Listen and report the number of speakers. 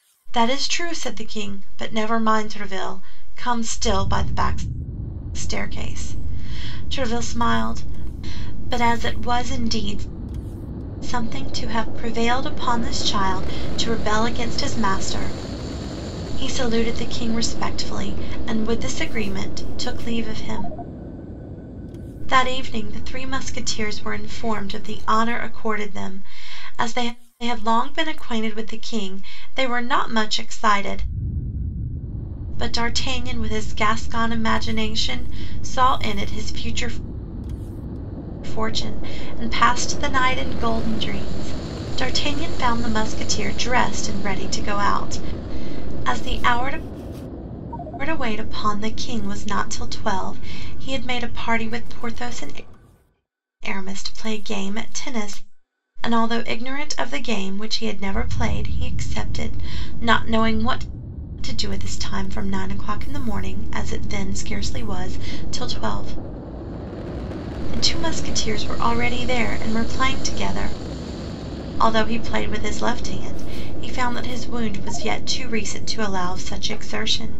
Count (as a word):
one